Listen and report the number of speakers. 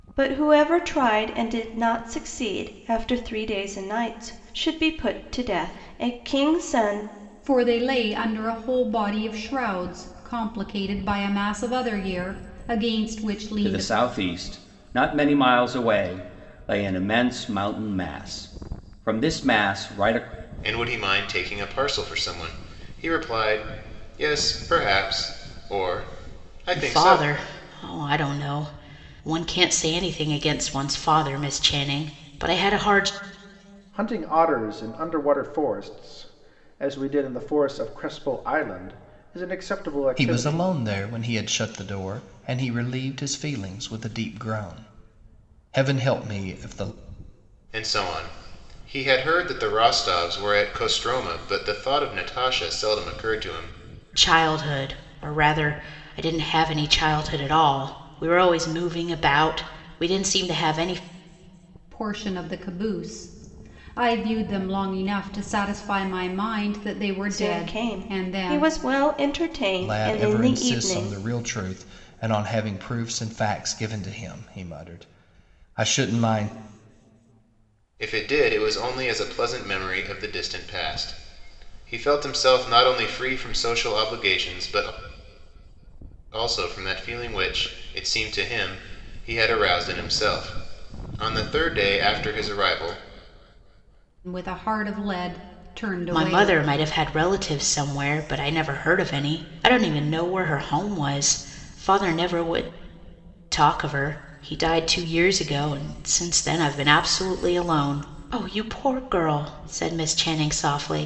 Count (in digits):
7